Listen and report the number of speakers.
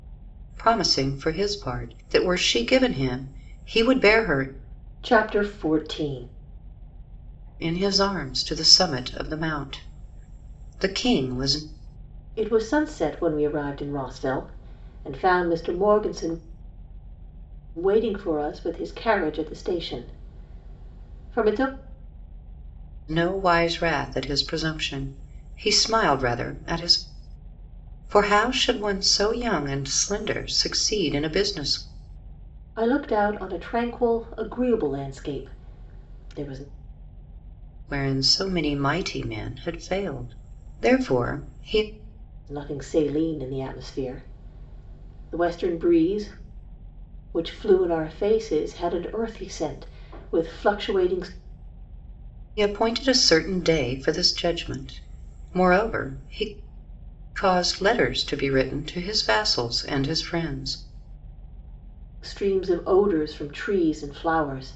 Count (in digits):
2